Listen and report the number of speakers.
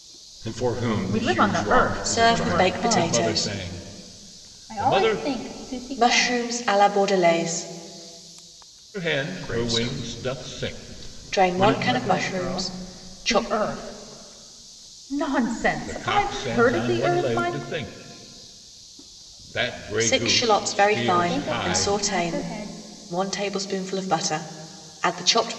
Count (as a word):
five